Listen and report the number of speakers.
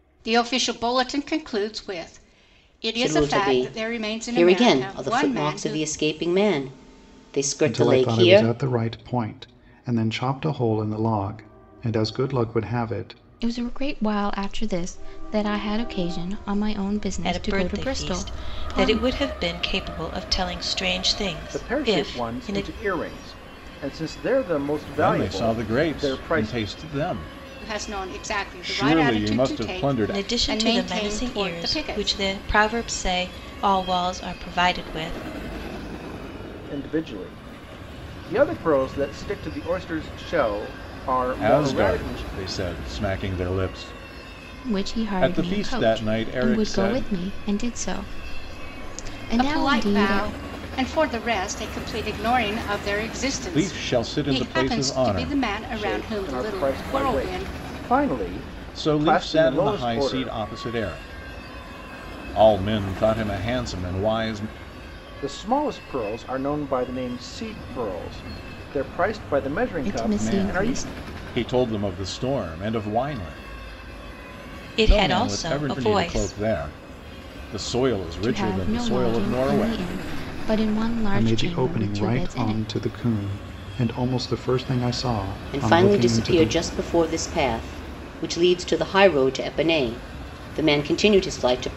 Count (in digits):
7